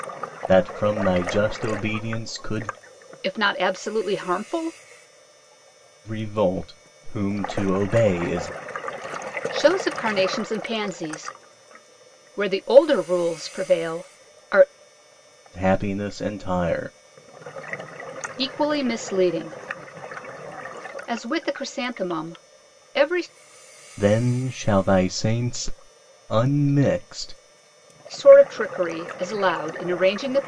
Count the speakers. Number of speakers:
two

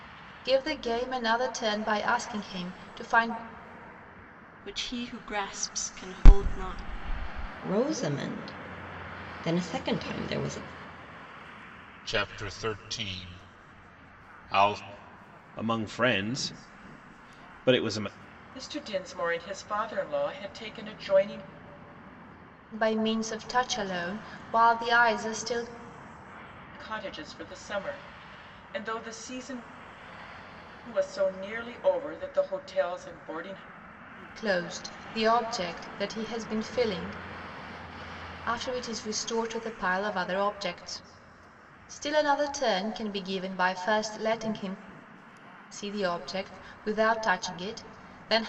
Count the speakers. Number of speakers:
six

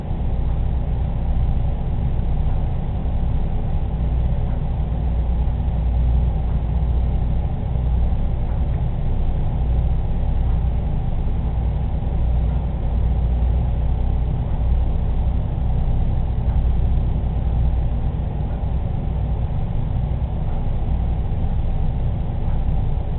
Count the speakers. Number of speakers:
zero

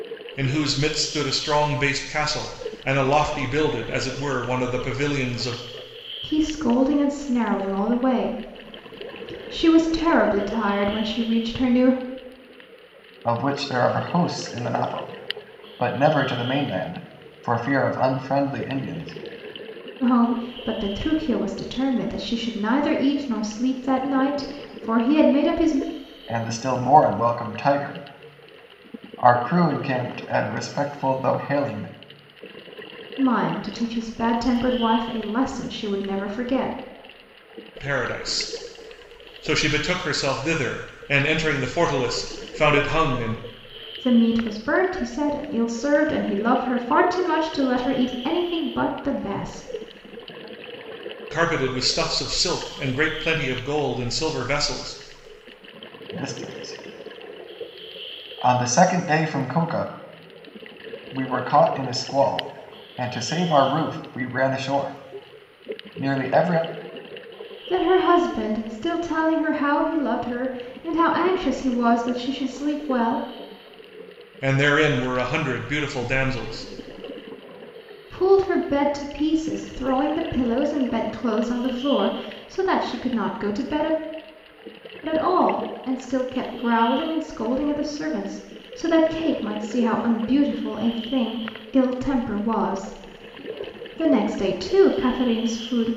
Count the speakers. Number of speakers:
three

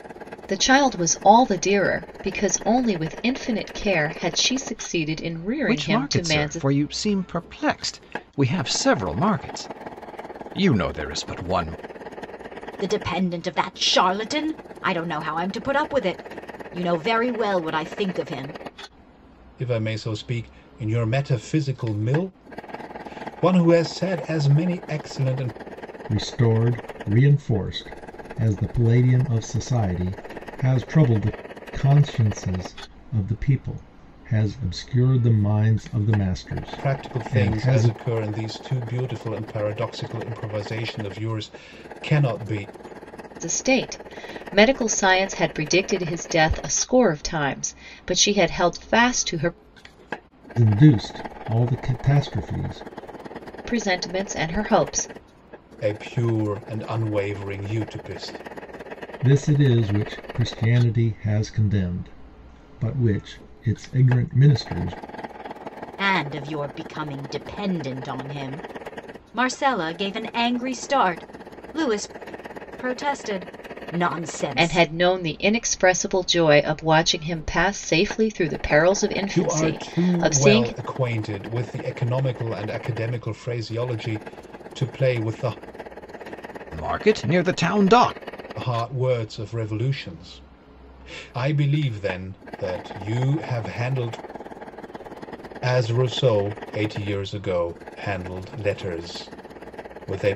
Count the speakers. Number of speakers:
five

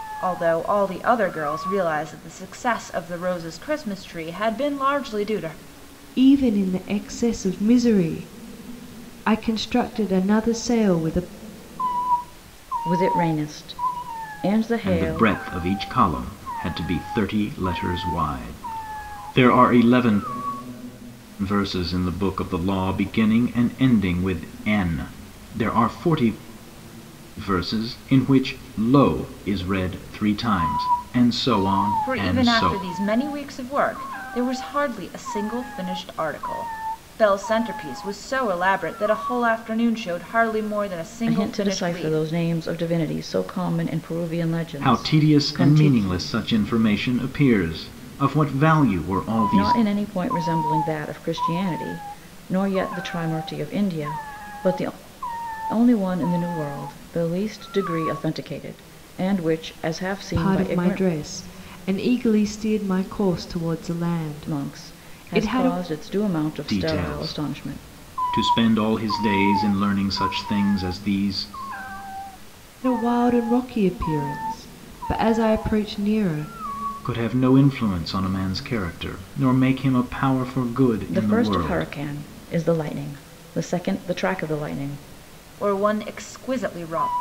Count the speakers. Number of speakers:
four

